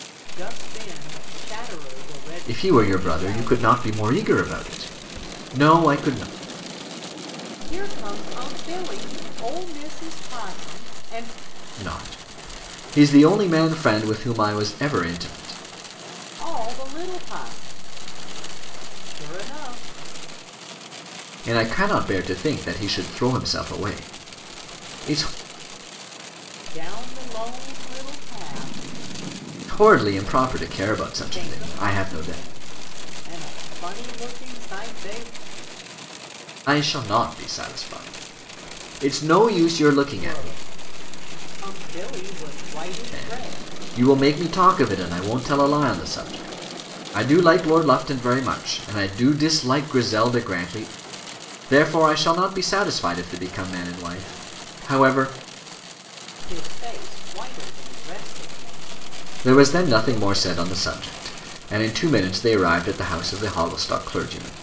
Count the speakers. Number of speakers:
two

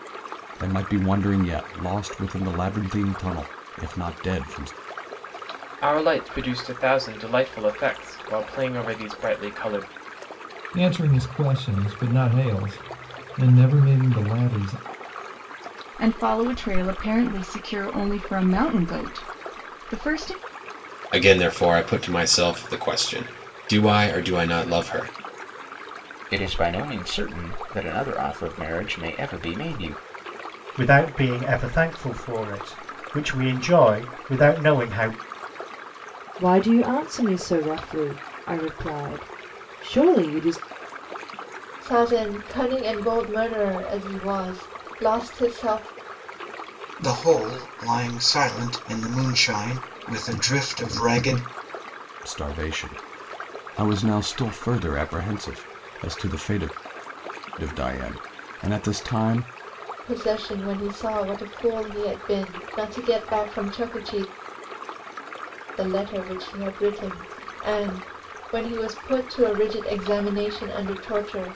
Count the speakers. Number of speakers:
ten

